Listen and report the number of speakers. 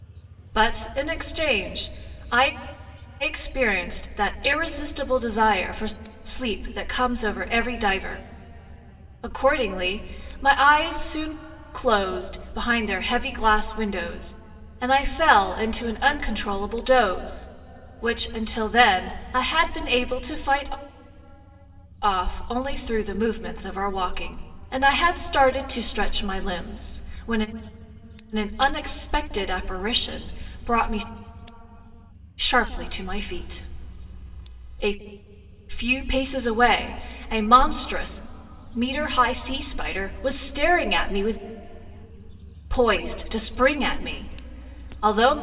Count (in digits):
1